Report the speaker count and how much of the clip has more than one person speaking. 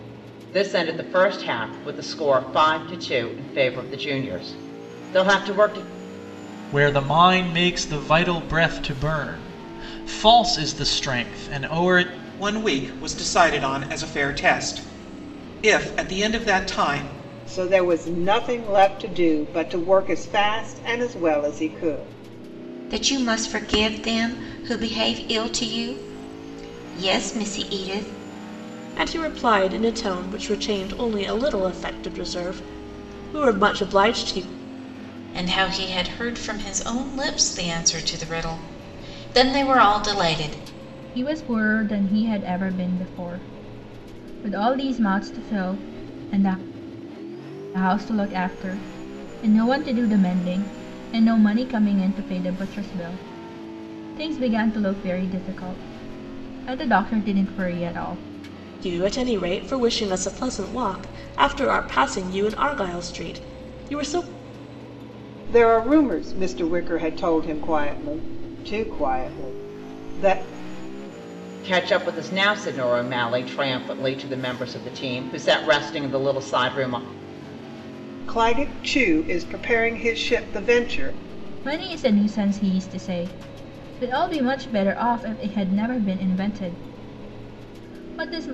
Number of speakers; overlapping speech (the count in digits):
8, no overlap